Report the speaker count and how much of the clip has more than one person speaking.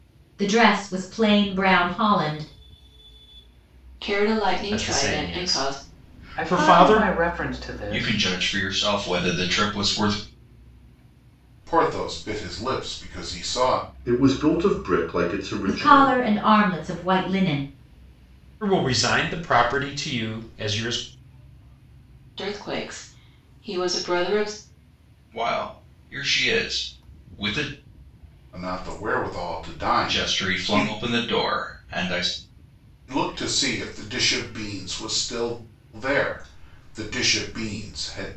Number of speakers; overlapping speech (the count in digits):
7, about 10%